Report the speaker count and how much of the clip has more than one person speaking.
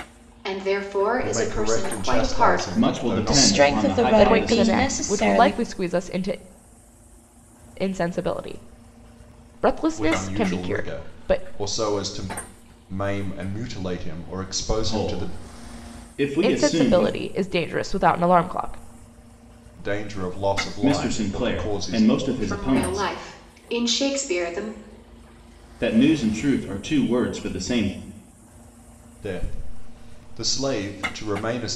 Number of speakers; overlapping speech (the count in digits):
5, about 30%